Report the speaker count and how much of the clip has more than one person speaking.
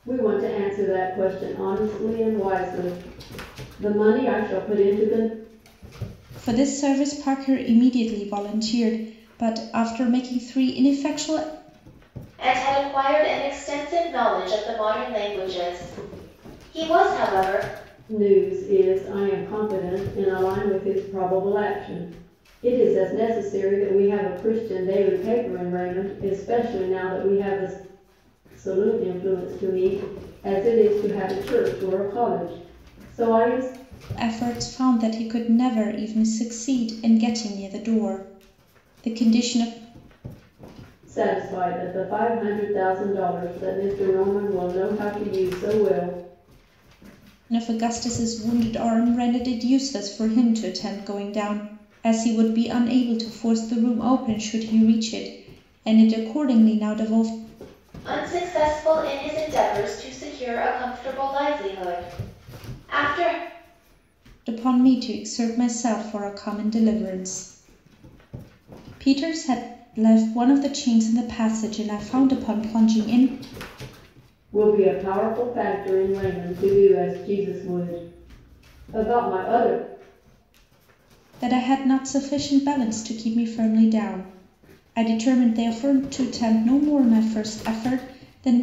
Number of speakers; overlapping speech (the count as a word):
three, no overlap